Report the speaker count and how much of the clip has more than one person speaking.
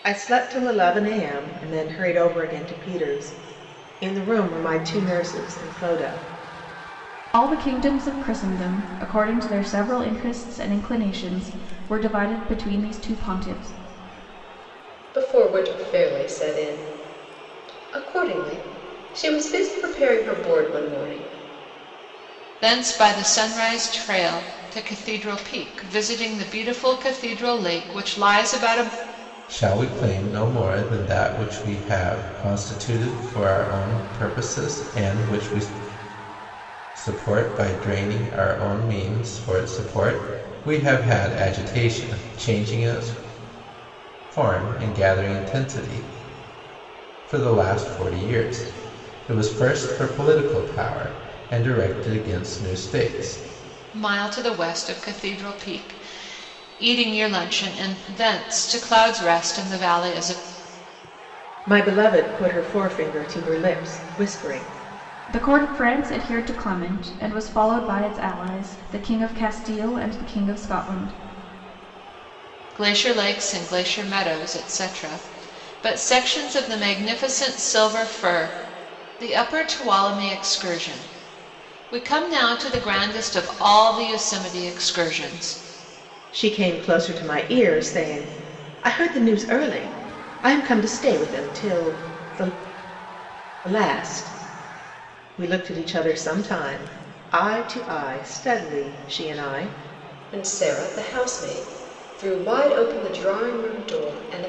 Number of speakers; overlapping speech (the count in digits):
5, no overlap